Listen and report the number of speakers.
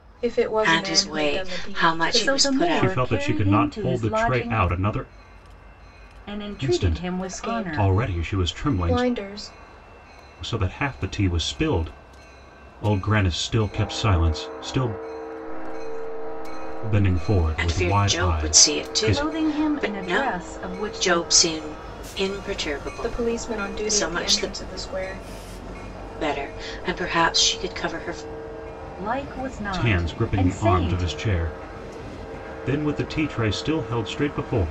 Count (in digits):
5